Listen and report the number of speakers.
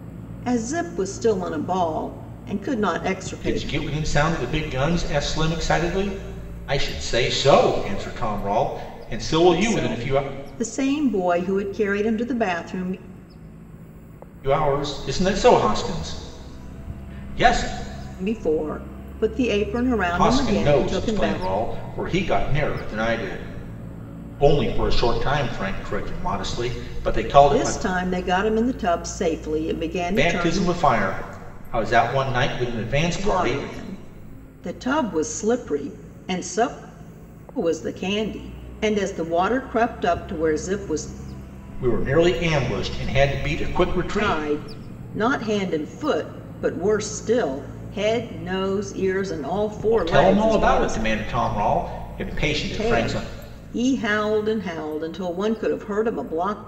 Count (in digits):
2